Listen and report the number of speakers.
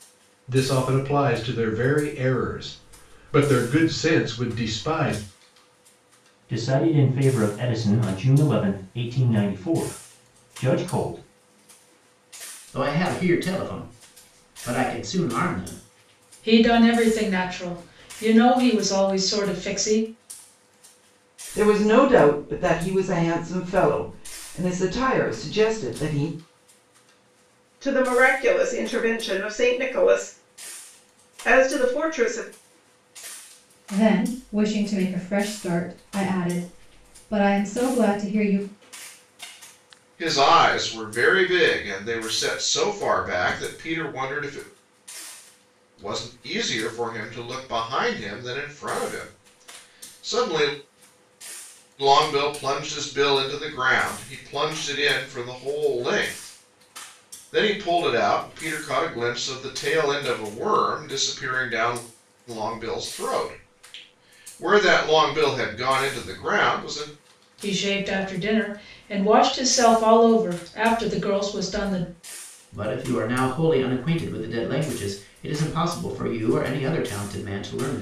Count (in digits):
8